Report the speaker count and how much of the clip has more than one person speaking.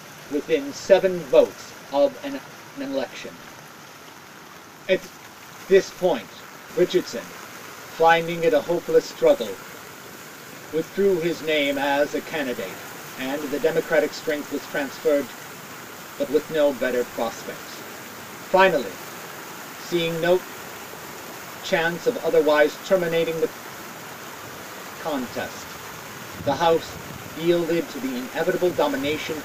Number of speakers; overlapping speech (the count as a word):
one, no overlap